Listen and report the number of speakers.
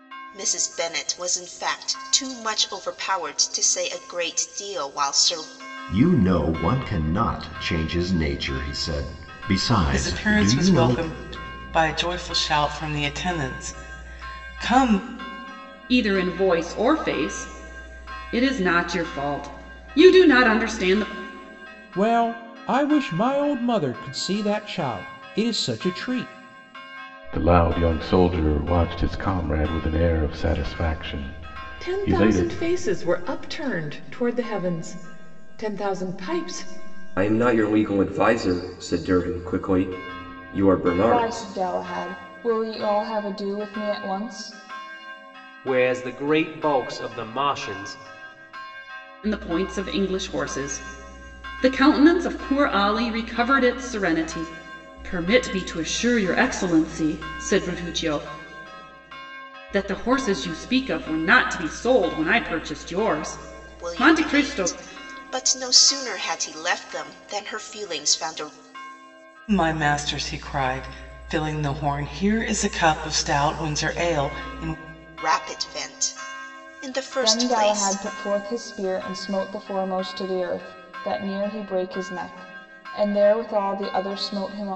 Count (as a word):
ten